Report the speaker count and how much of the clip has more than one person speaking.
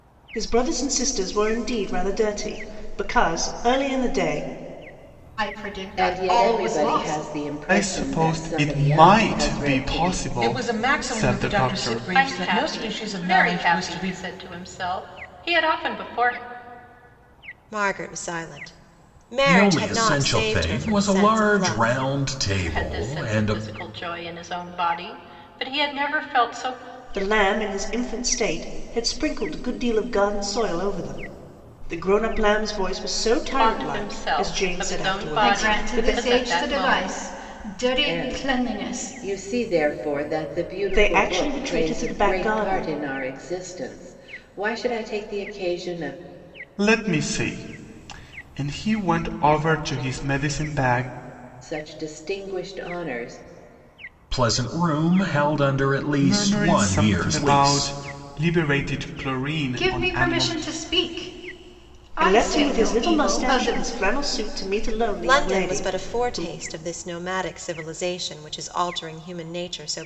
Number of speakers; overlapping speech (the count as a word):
eight, about 34%